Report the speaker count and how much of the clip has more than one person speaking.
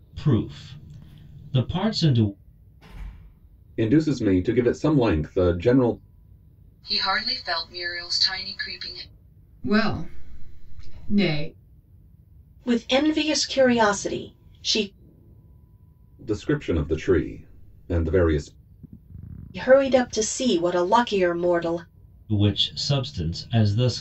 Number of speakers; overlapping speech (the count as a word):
five, no overlap